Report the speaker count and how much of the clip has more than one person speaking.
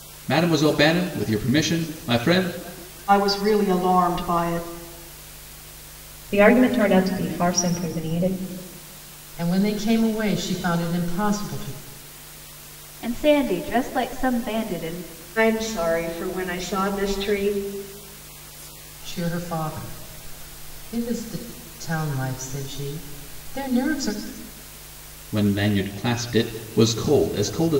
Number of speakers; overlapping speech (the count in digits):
6, no overlap